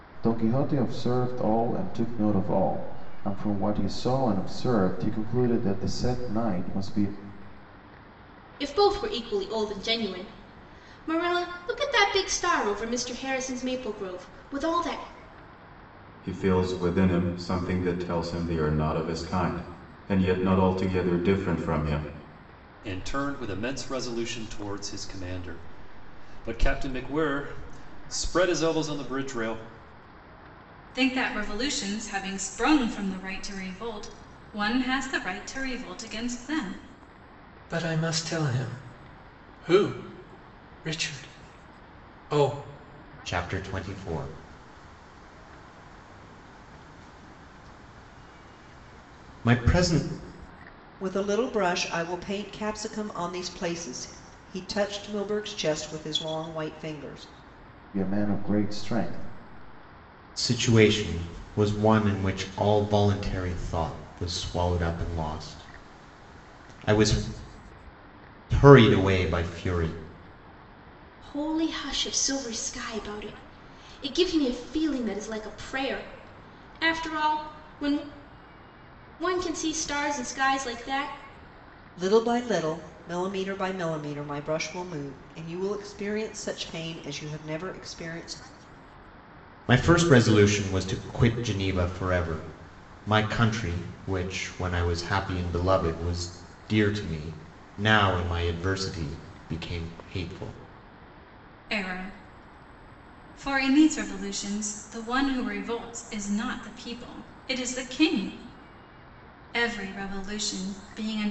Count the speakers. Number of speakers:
eight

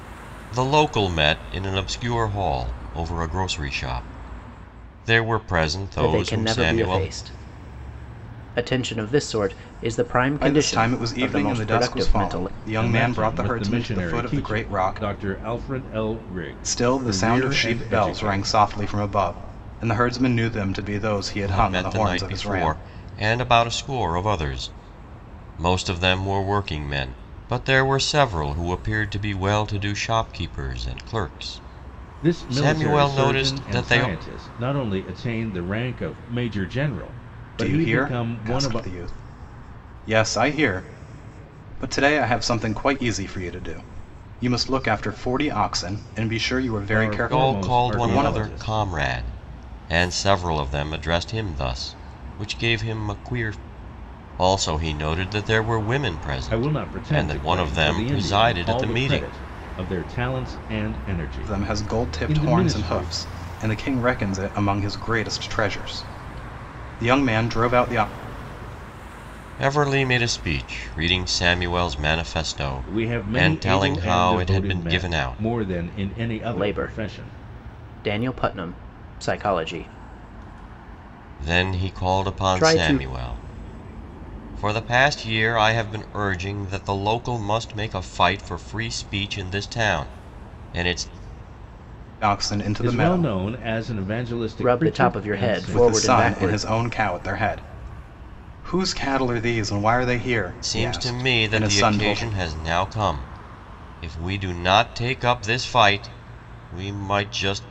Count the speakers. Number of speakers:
four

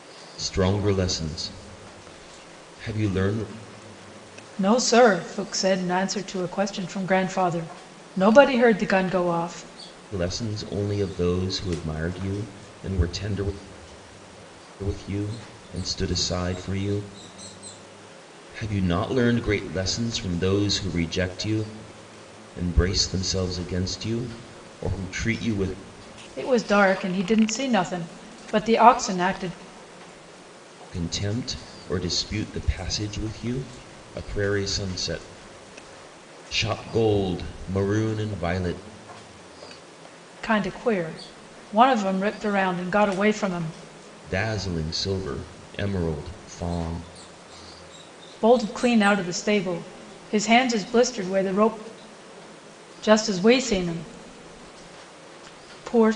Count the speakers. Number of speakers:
two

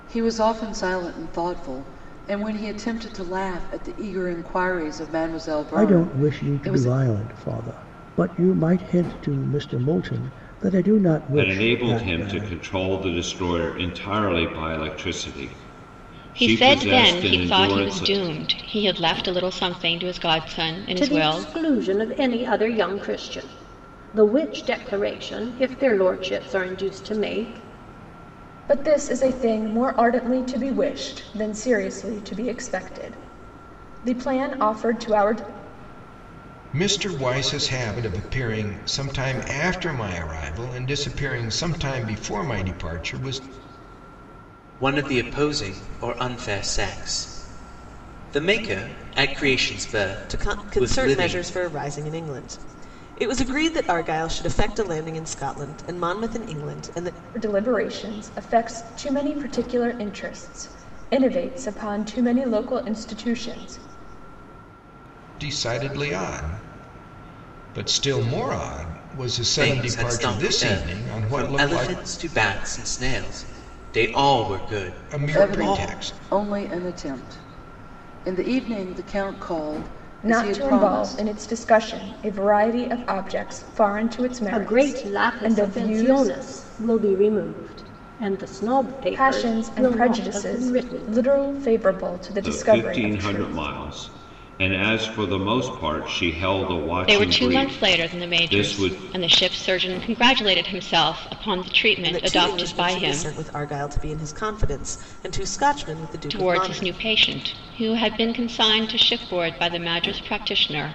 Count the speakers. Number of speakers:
nine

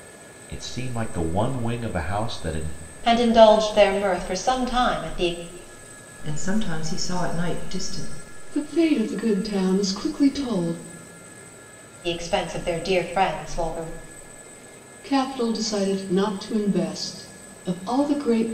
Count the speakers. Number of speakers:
four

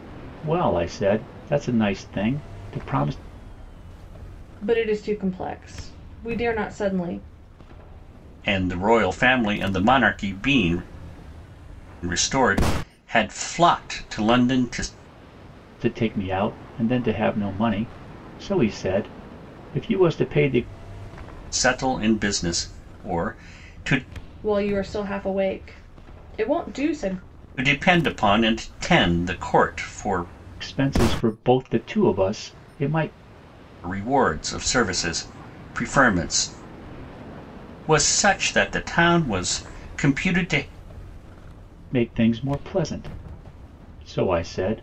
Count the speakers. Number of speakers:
three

